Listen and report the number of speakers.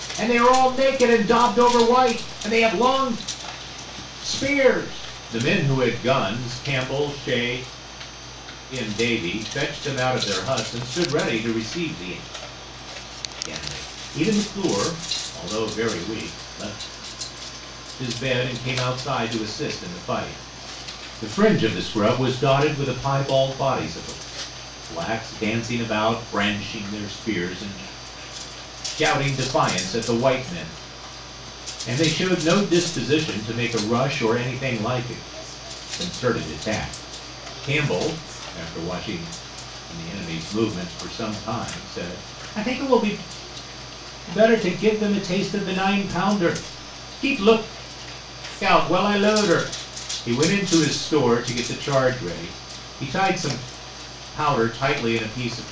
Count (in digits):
1